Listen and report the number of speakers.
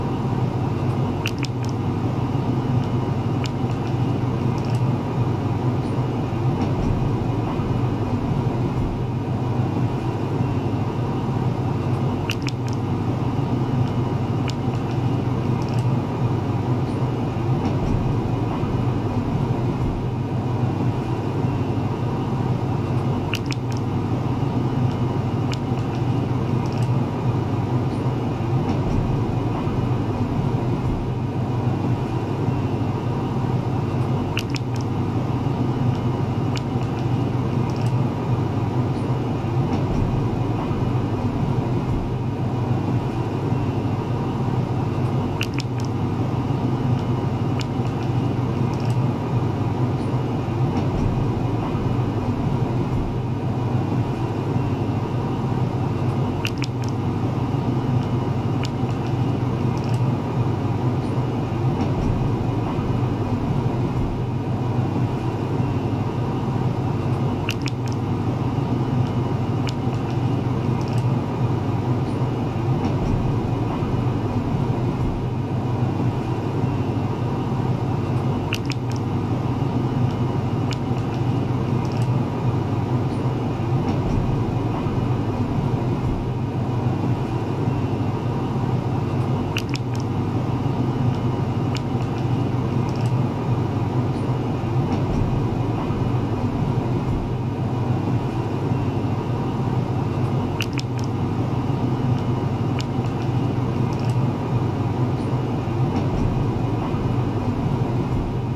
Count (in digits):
0